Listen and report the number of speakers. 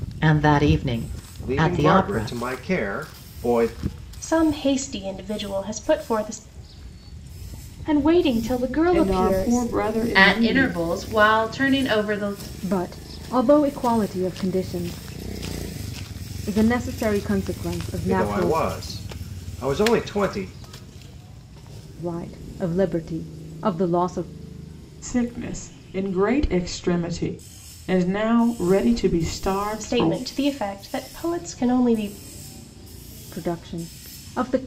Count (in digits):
7